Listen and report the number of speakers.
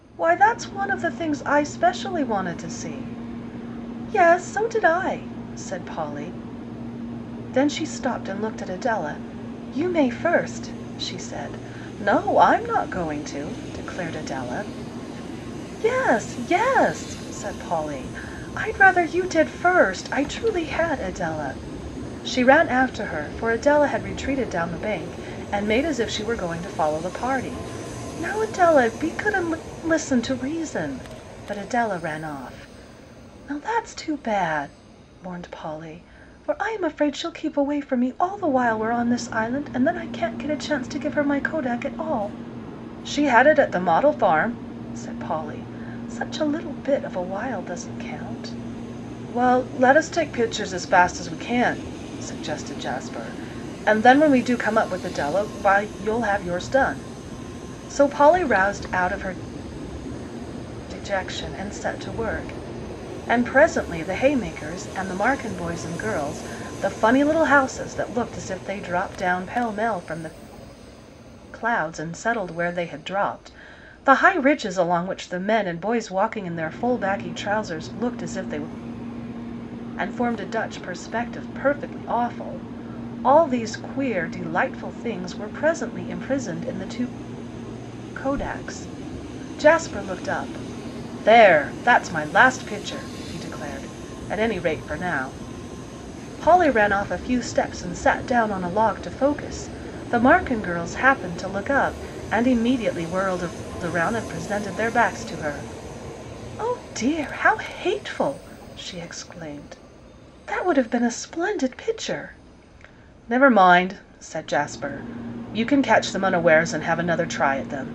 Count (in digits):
1